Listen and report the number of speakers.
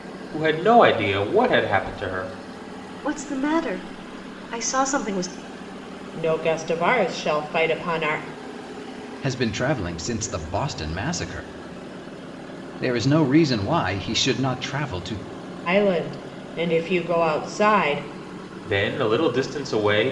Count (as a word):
four